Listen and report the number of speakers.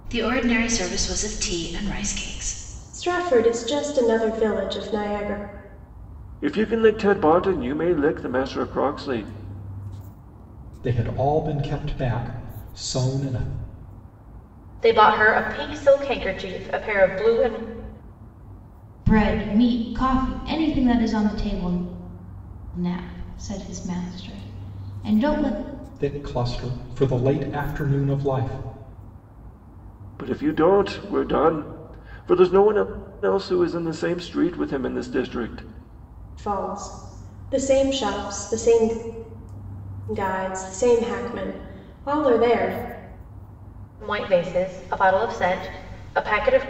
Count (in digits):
6